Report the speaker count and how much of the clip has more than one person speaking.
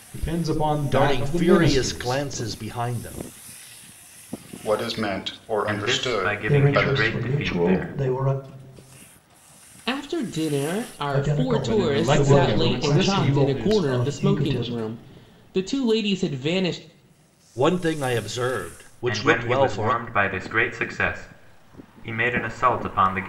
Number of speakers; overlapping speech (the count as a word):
six, about 36%